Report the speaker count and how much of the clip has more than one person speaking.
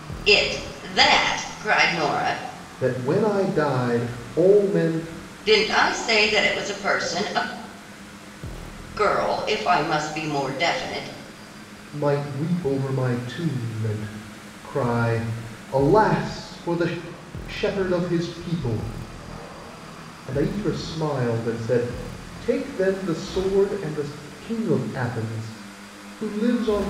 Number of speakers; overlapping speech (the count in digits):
2, no overlap